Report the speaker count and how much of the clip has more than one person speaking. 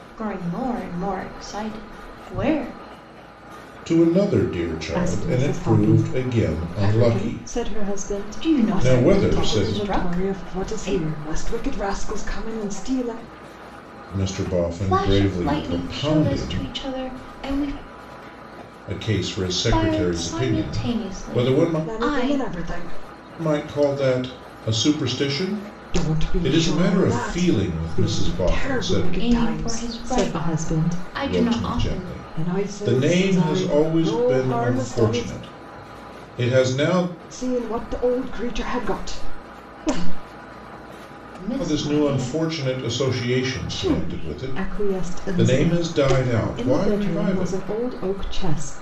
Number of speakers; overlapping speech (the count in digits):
3, about 47%